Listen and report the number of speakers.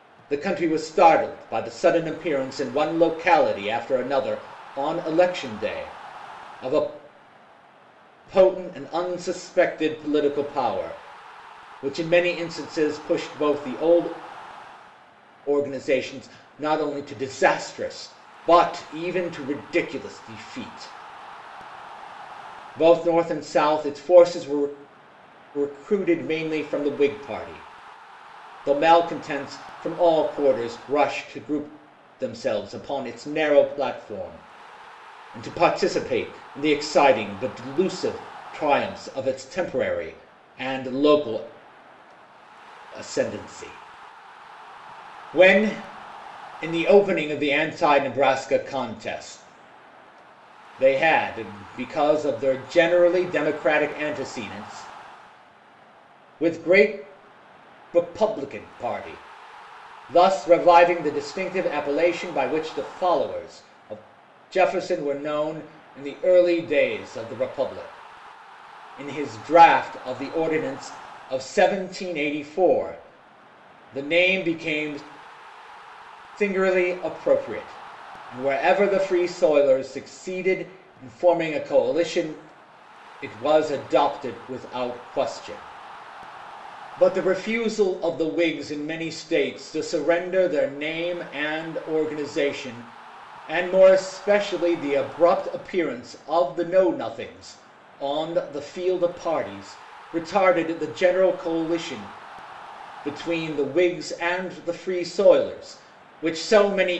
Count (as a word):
one